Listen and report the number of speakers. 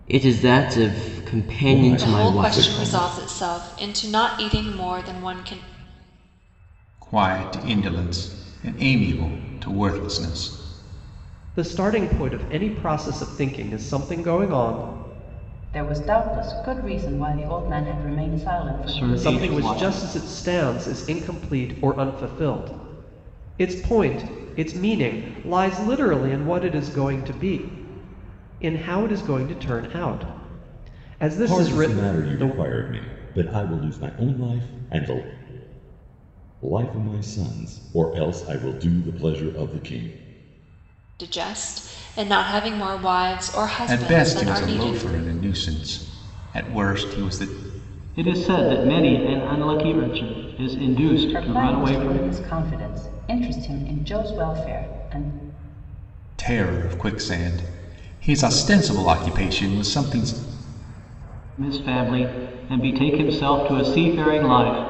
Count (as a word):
seven